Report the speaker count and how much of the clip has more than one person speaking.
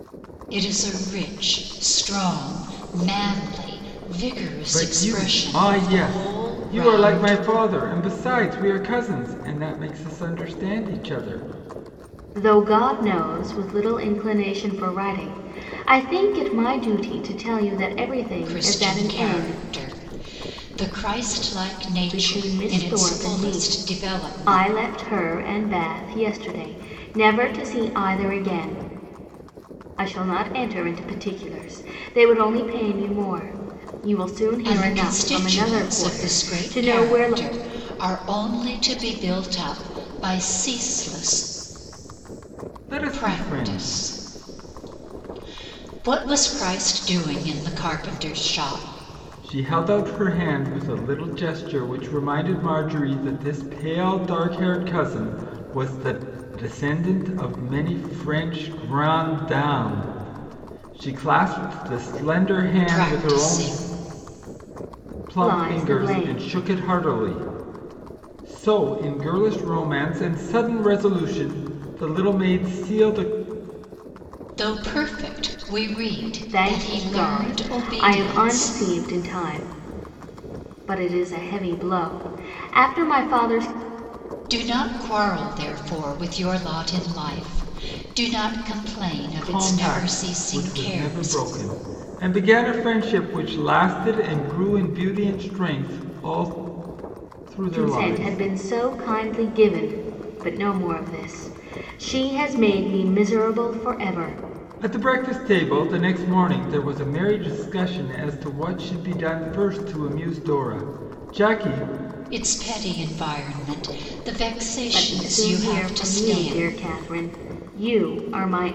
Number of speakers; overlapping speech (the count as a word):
three, about 16%